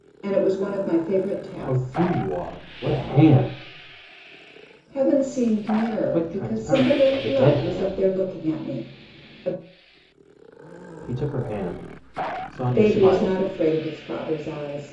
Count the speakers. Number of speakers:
2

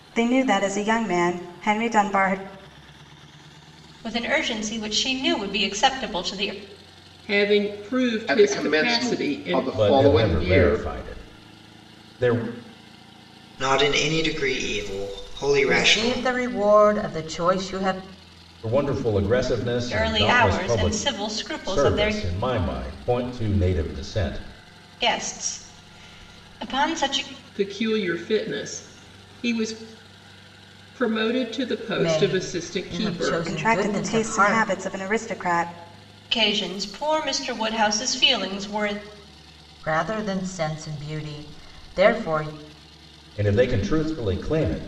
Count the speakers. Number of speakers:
7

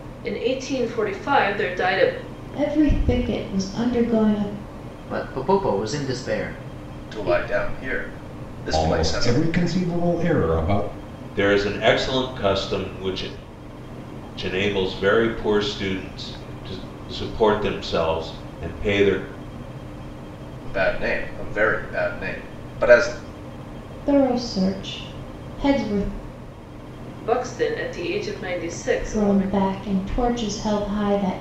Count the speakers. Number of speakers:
6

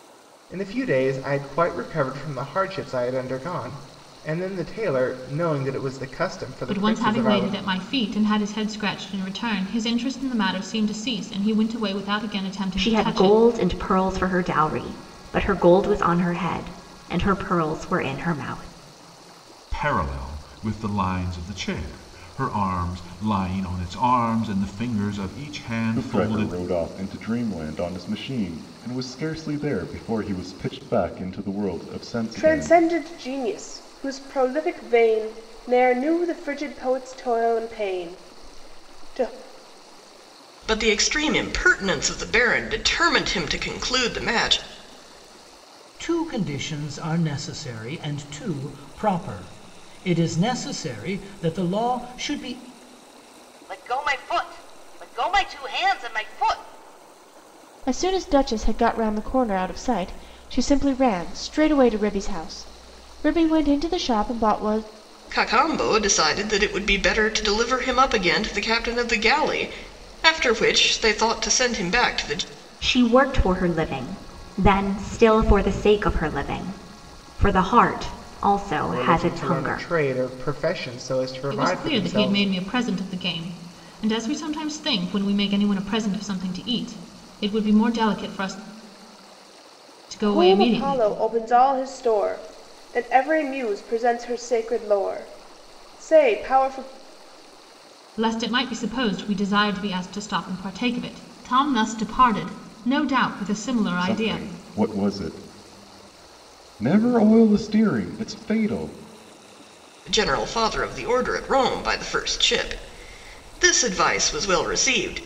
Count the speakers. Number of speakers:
10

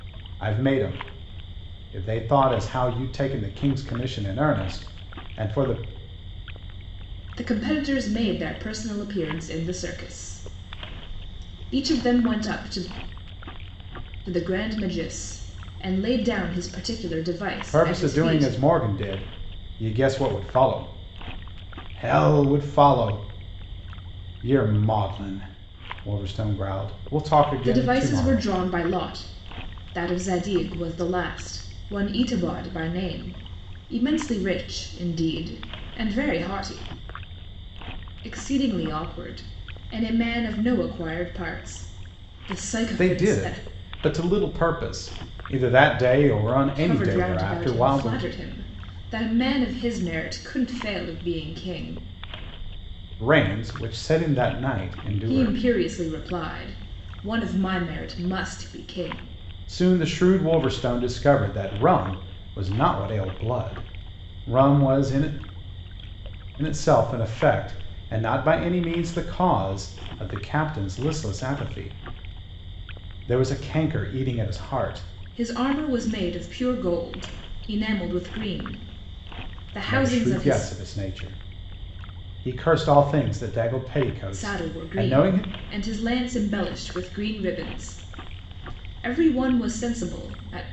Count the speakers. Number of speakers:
2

